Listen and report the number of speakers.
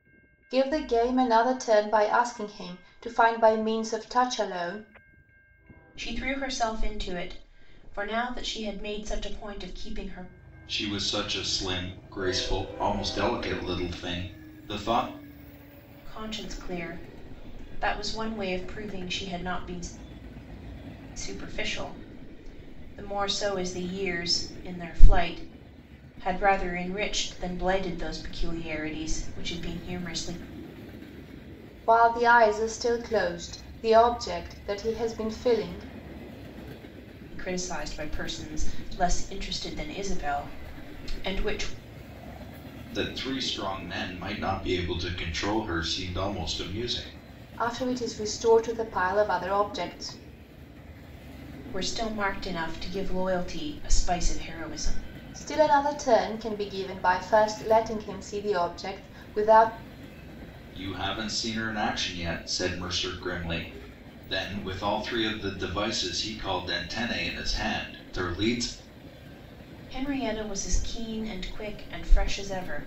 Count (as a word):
three